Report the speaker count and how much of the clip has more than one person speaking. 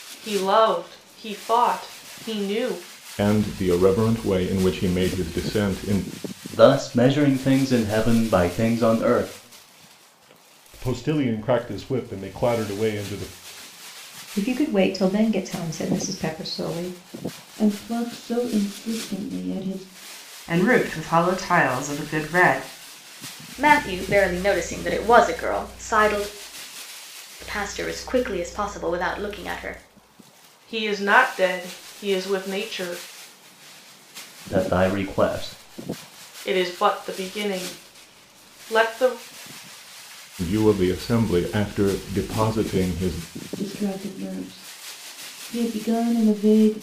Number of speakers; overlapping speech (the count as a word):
eight, no overlap